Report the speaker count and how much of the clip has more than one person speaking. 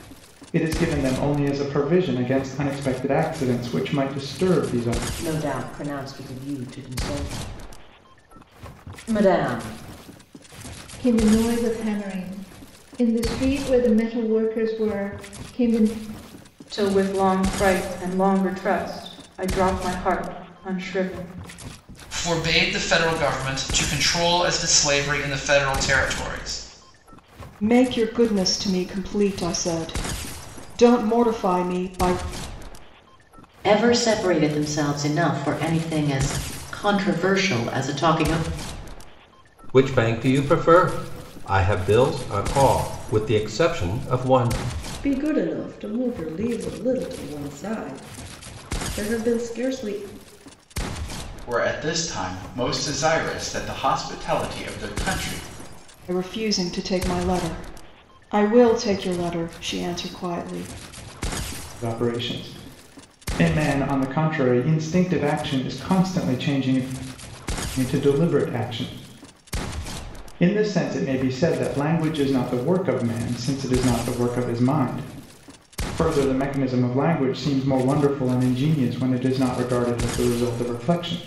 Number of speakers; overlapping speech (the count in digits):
10, no overlap